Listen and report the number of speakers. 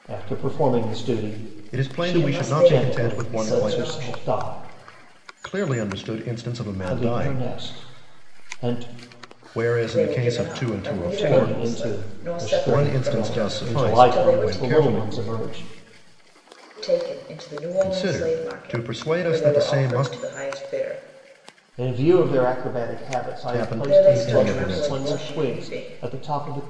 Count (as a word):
three